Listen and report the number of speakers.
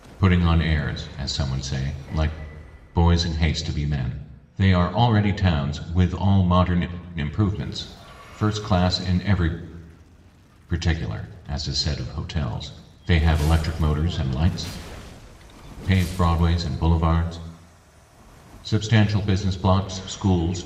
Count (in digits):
1